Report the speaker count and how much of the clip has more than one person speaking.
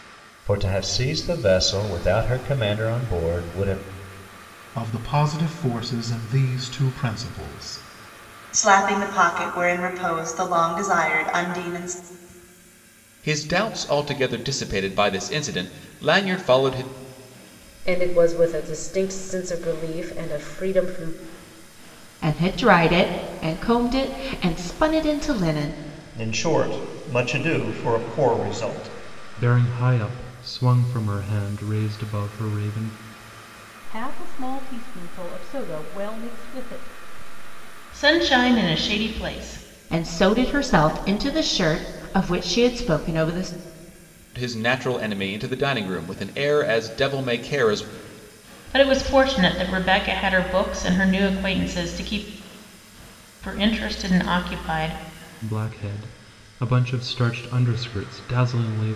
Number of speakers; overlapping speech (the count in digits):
10, no overlap